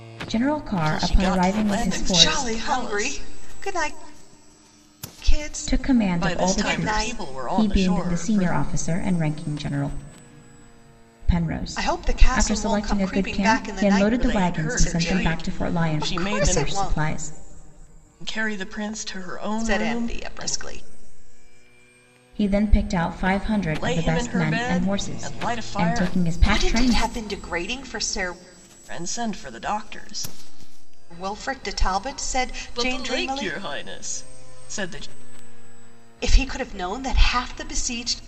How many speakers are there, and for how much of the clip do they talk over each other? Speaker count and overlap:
3, about 41%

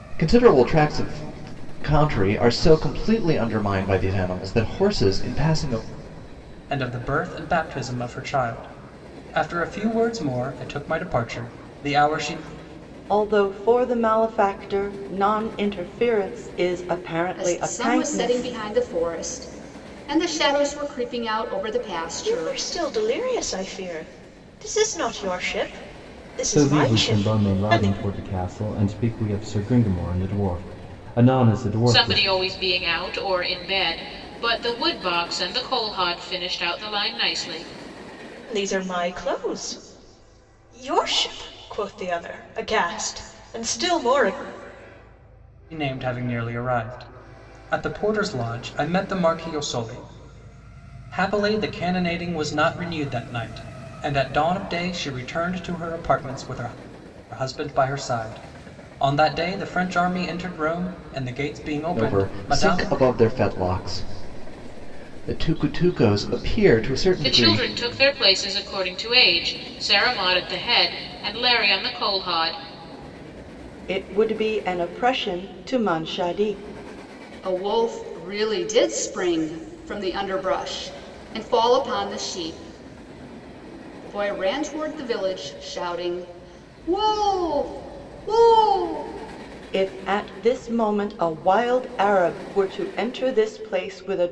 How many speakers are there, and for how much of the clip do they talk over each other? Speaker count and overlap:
7, about 5%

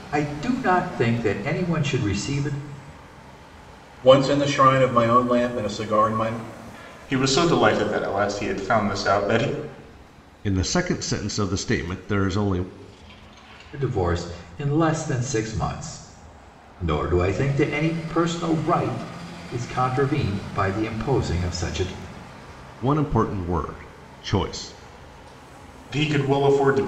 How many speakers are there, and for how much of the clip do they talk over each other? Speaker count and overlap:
4, no overlap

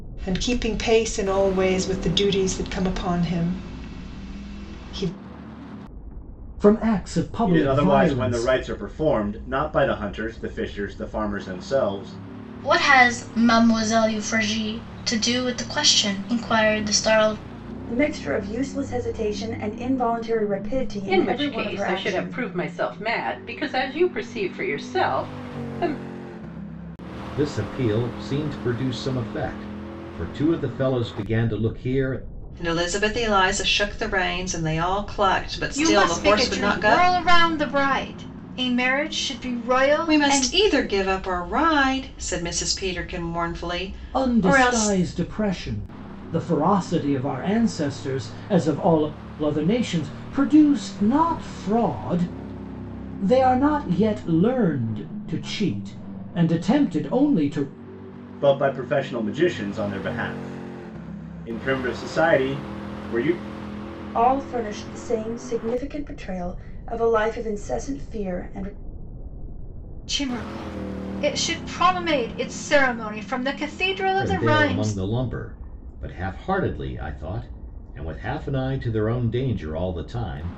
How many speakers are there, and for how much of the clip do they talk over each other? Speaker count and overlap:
9, about 7%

